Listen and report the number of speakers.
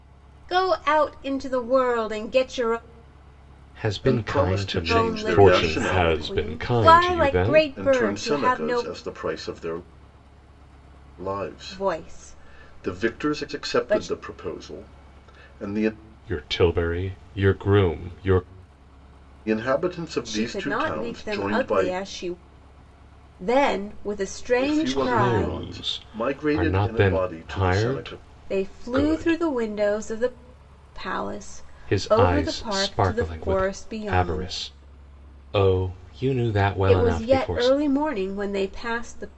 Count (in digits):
3